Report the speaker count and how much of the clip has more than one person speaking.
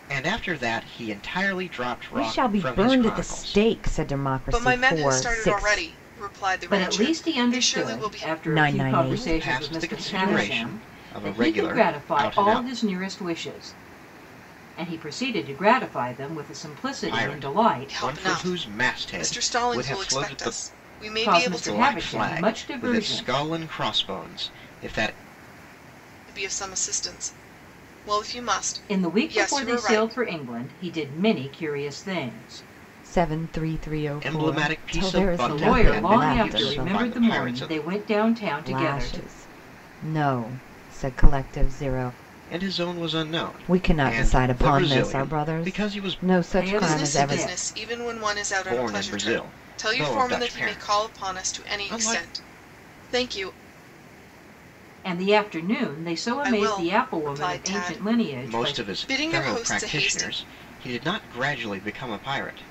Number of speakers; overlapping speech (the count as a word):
four, about 50%